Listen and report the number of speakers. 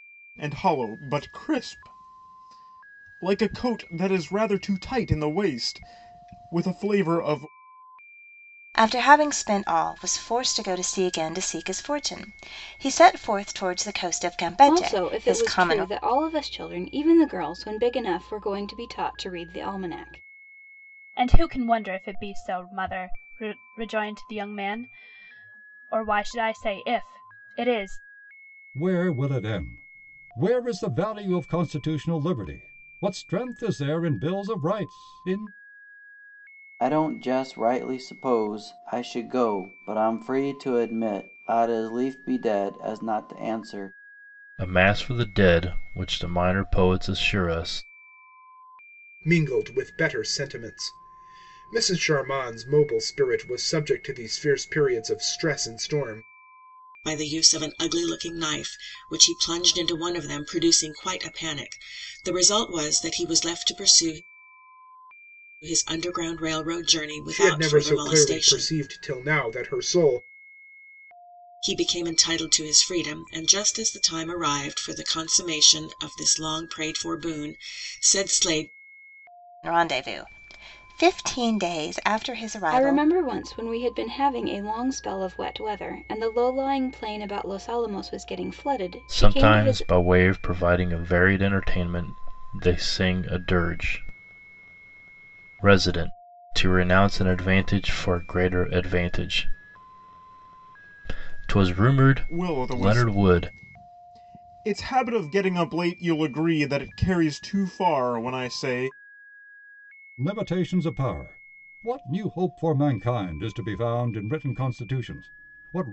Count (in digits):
9